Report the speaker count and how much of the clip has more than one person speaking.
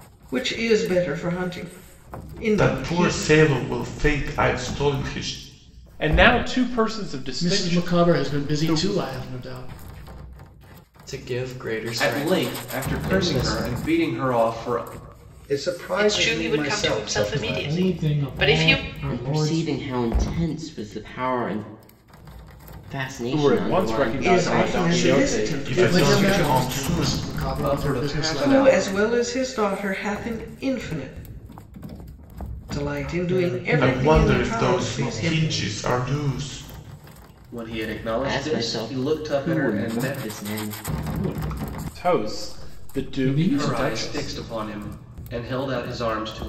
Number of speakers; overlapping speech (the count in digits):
10, about 42%